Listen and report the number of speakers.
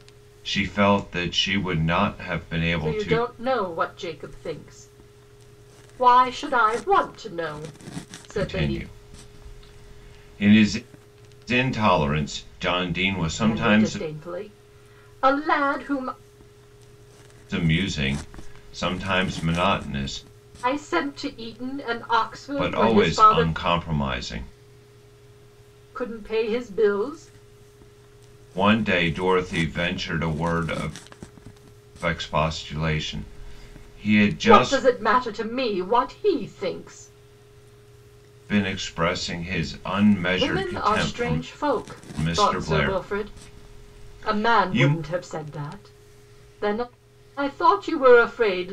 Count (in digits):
2